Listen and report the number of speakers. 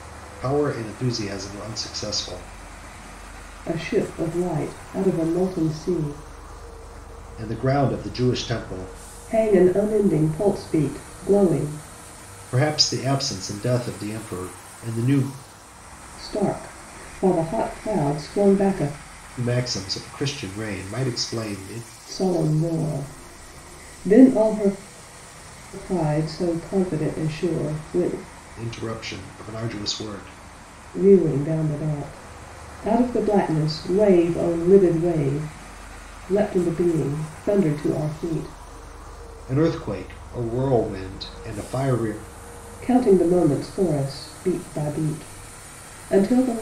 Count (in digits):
2